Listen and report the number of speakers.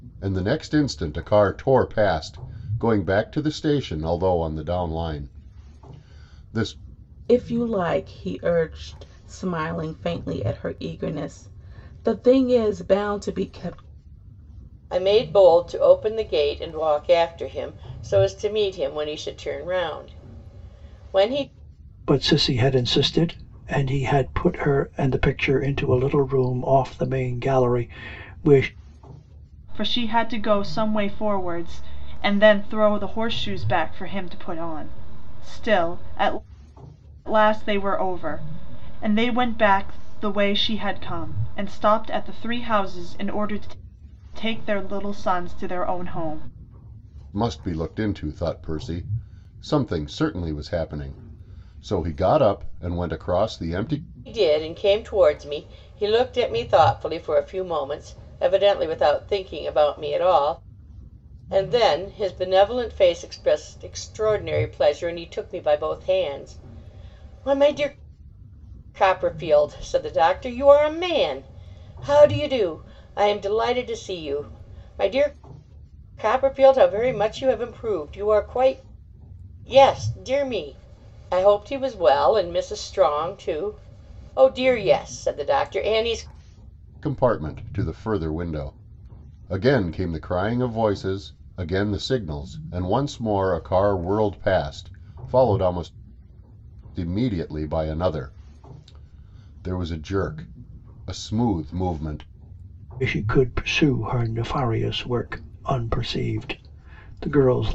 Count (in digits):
5